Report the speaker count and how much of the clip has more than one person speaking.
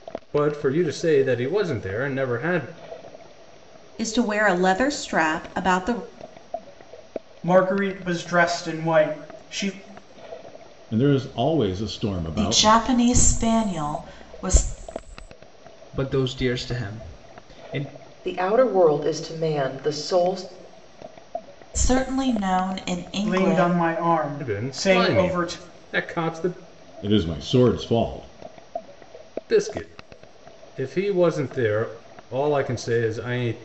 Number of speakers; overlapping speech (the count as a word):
seven, about 7%